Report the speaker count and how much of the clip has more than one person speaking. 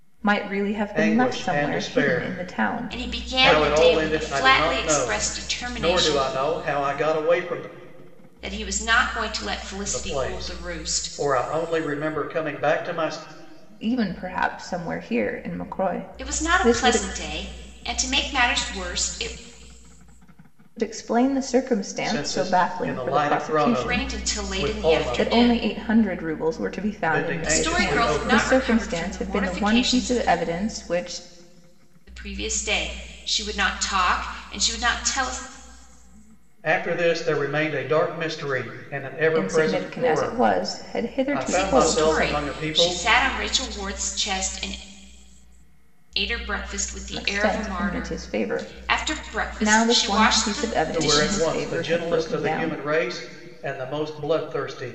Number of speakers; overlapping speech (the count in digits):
3, about 43%